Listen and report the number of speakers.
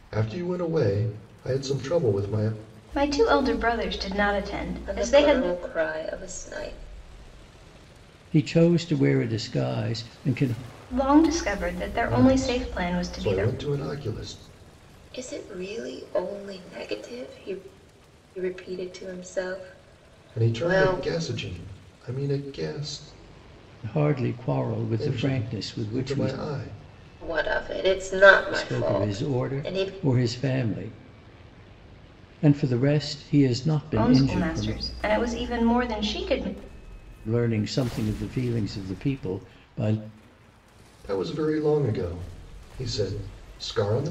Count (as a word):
four